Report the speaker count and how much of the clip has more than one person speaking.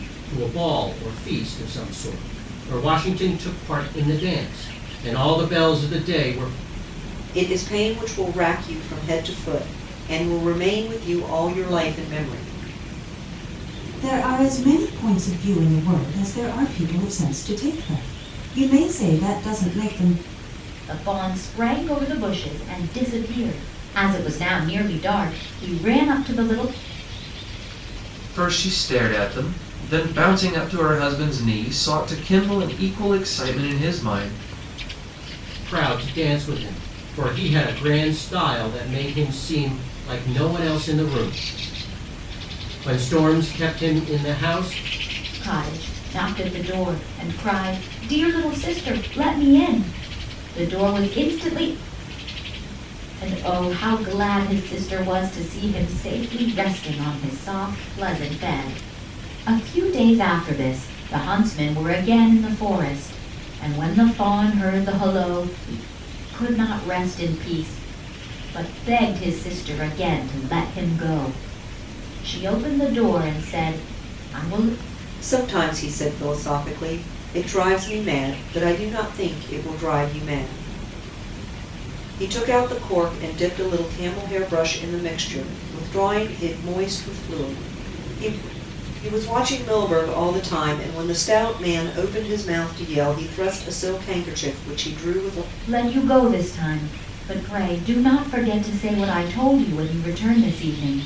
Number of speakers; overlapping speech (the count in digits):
5, no overlap